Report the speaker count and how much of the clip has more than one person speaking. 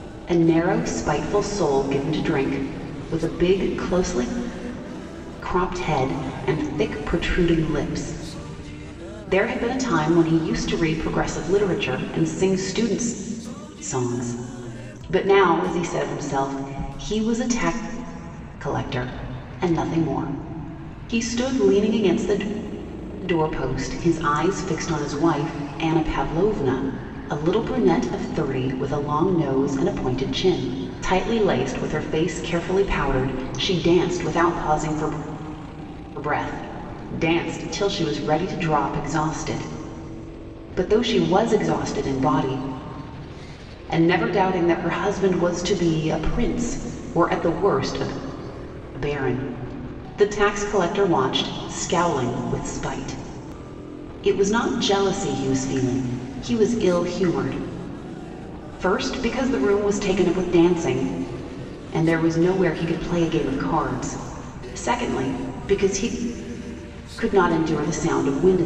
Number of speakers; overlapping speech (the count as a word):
one, no overlap